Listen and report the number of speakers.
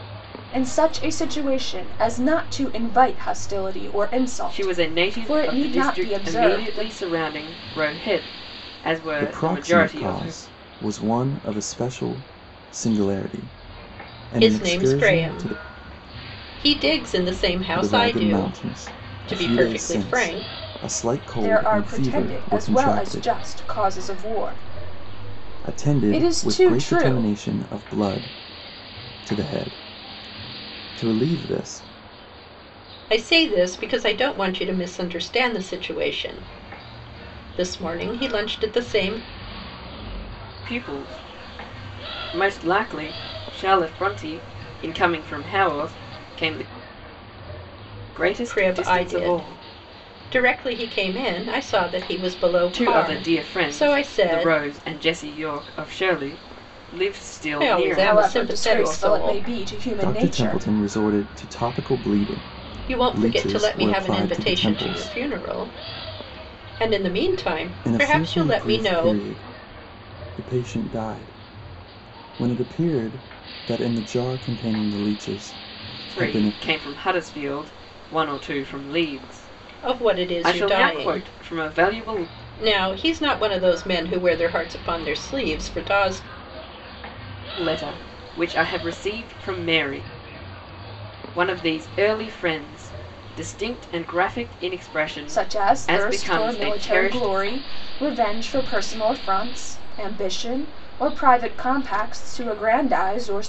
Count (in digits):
4